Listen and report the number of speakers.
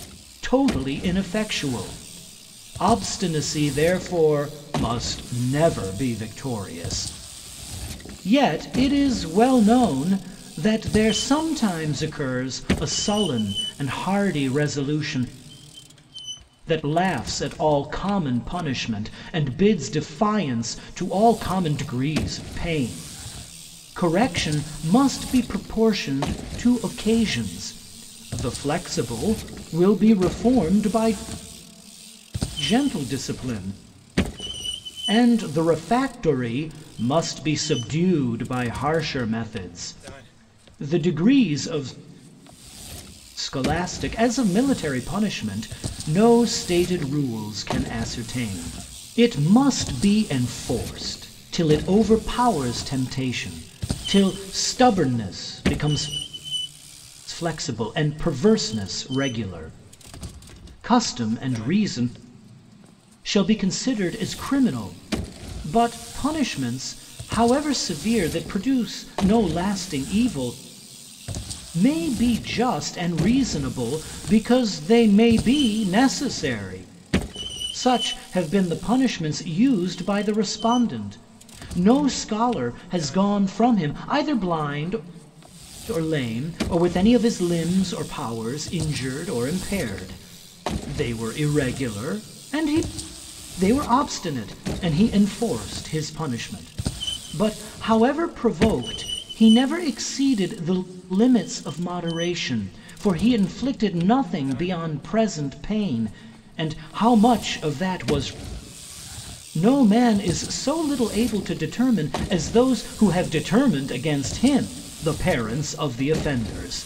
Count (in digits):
1